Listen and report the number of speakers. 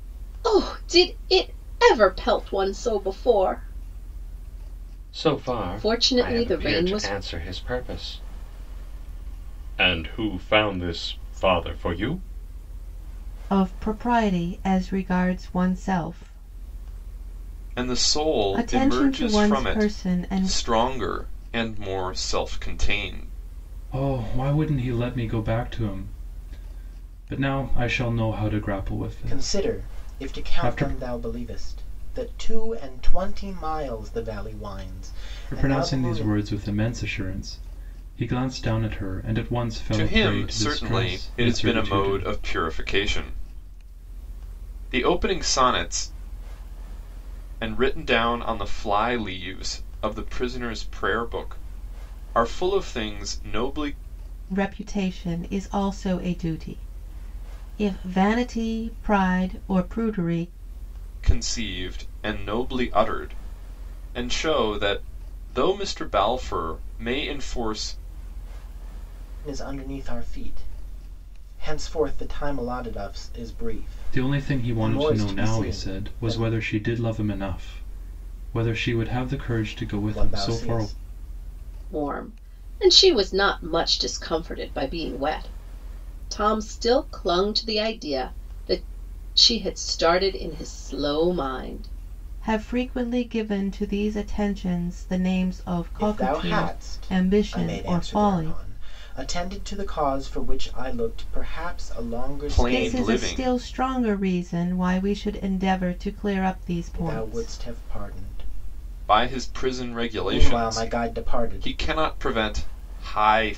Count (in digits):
6